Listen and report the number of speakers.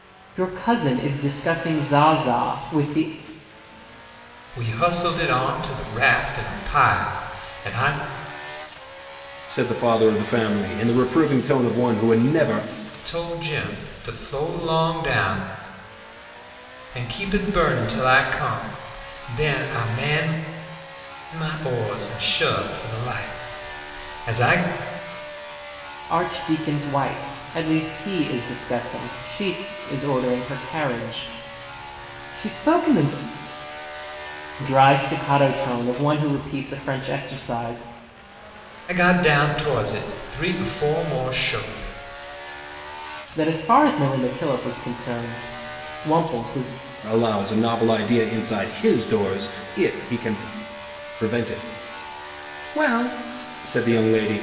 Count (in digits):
3